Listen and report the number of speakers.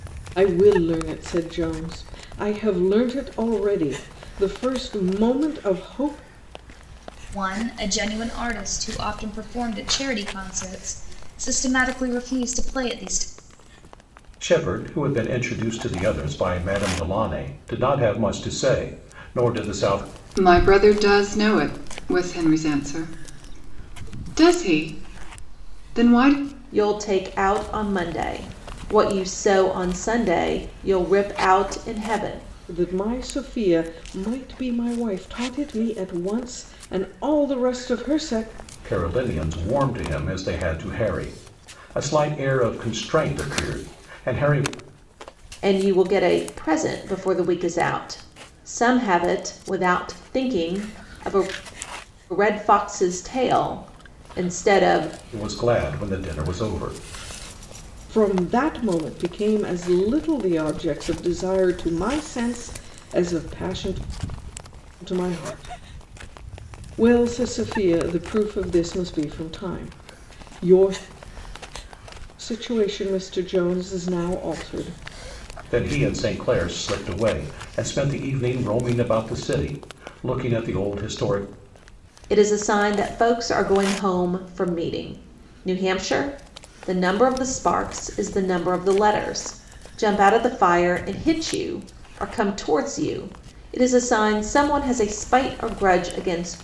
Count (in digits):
5